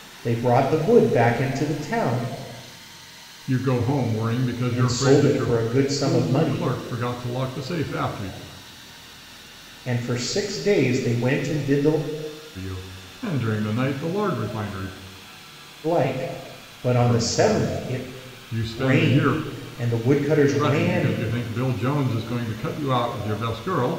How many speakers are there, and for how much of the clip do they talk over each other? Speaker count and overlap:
two, about 17%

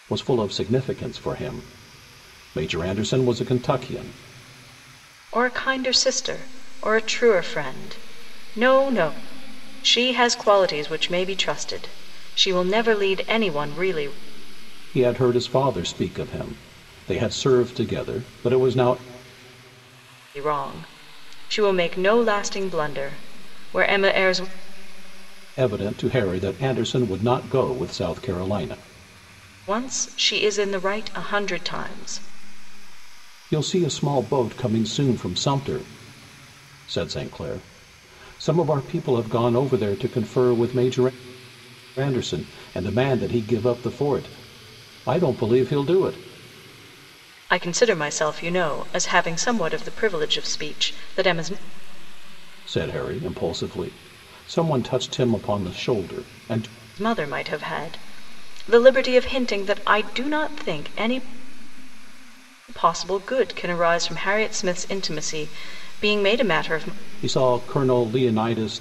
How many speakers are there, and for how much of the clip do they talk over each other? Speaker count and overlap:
two, no overlap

